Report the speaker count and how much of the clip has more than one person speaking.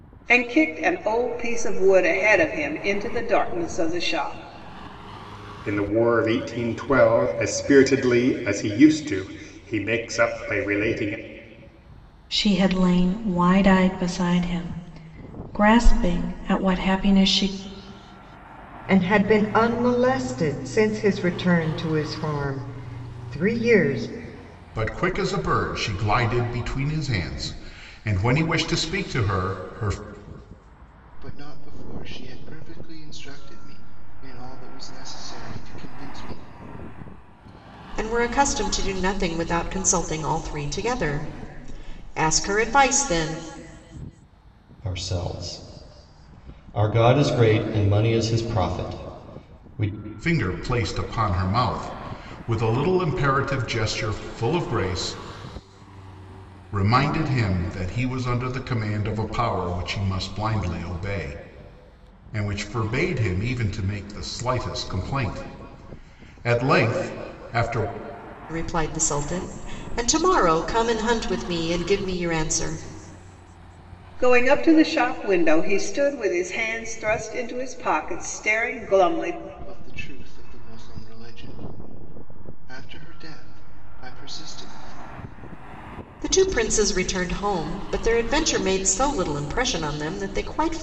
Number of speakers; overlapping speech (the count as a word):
eight, no overlap